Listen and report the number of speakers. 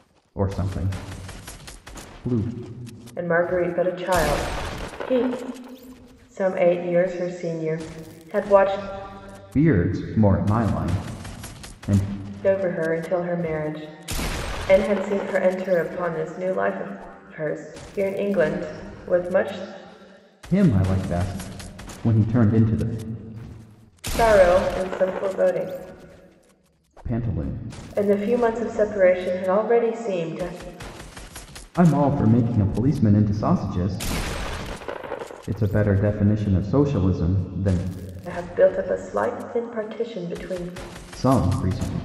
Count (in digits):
2